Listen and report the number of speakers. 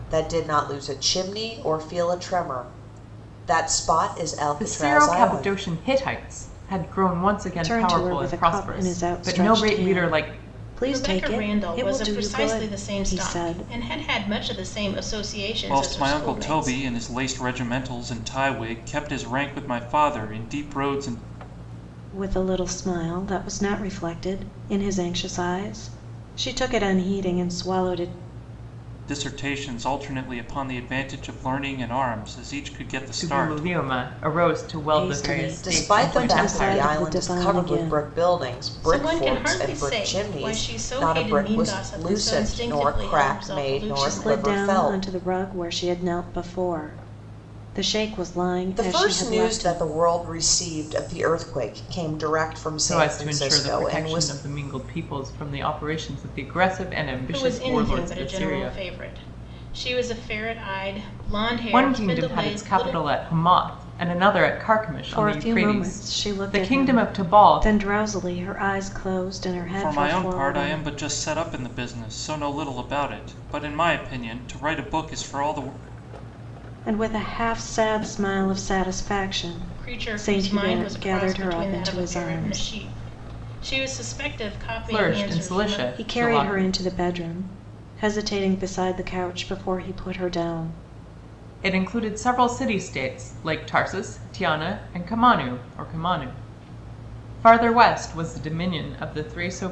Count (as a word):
five